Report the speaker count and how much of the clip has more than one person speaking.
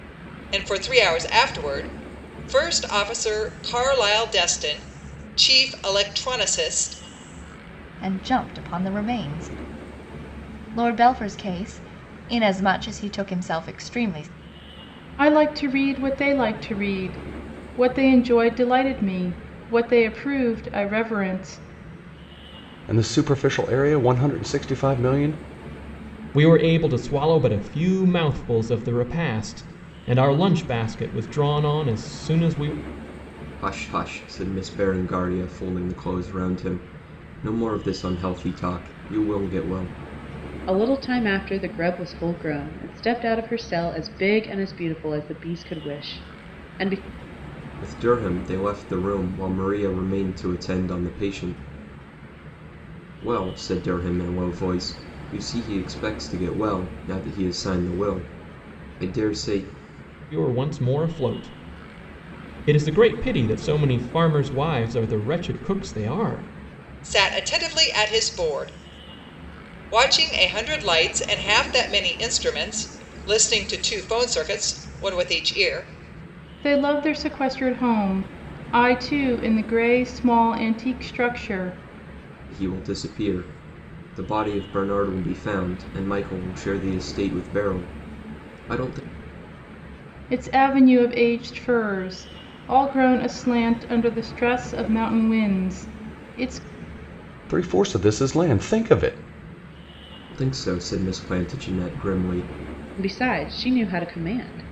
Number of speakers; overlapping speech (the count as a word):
seven, no overlap